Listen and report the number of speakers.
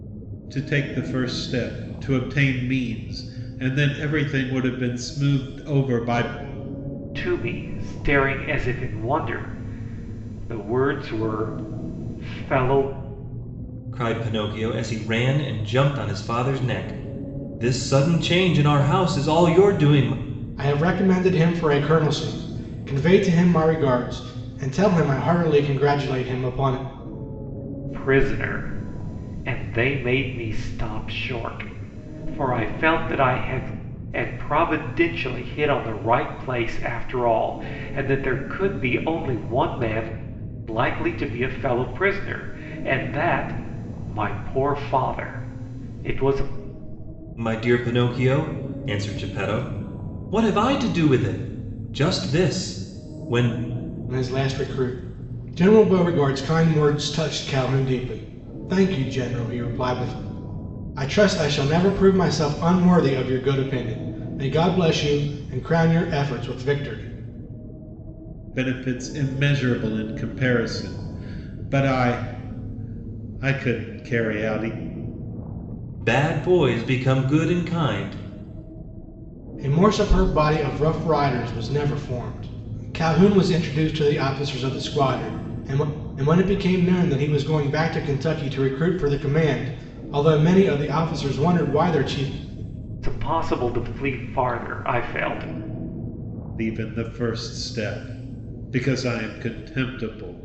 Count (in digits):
4